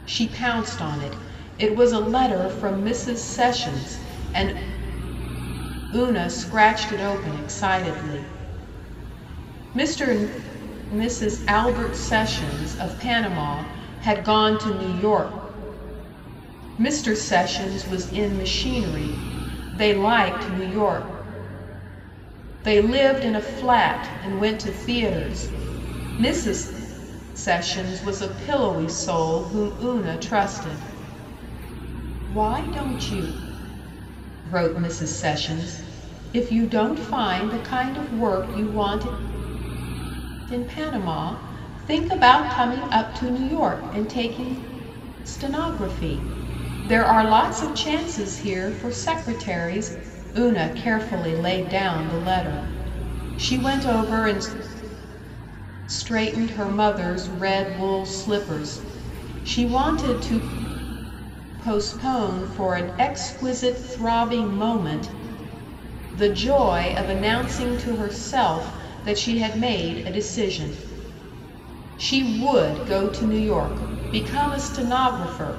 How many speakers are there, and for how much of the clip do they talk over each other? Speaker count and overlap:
one, no overlap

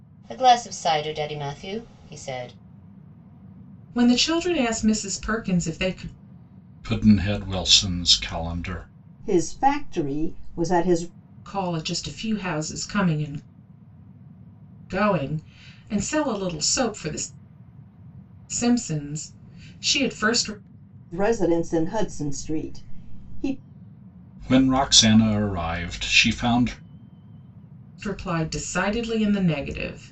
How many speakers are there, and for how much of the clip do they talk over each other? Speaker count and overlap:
four, no overlap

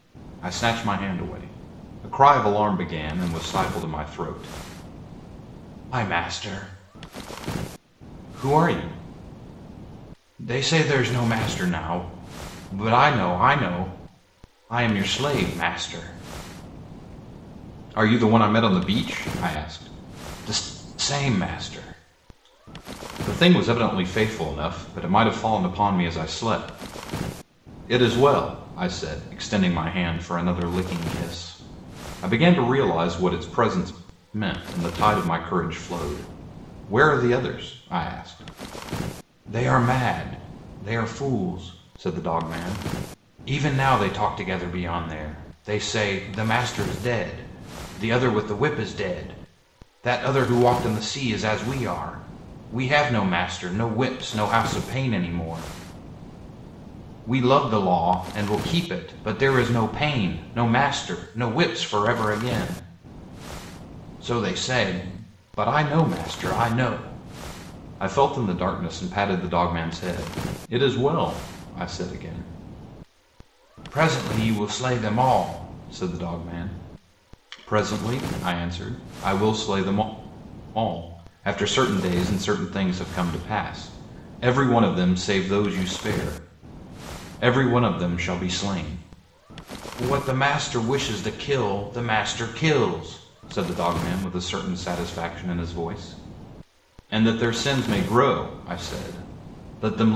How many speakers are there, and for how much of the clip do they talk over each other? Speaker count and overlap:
one, no overlap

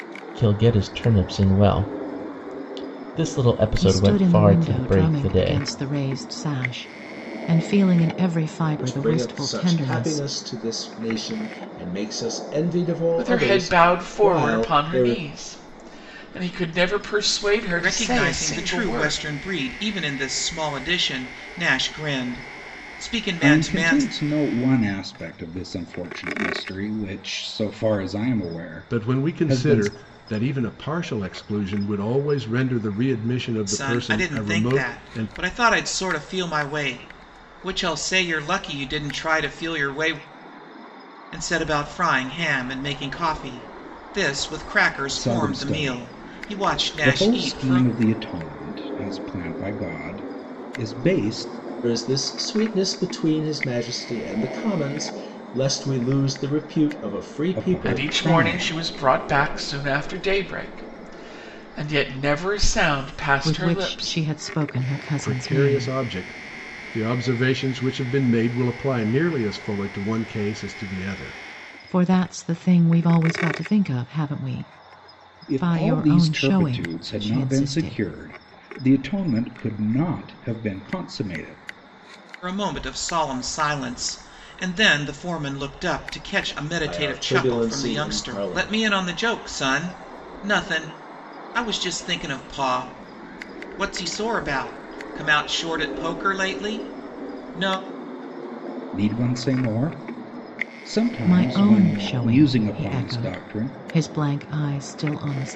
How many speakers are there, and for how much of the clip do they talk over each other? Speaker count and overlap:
seven, about 22%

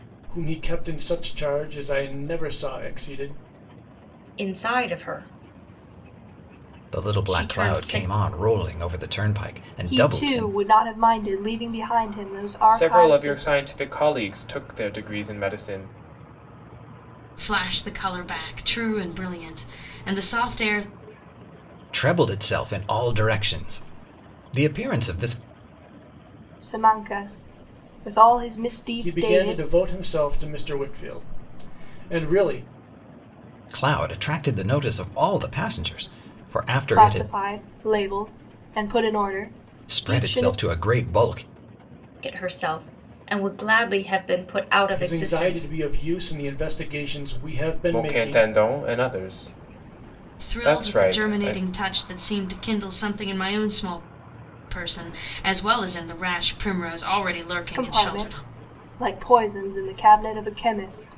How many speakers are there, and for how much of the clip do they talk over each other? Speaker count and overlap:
six, about 14%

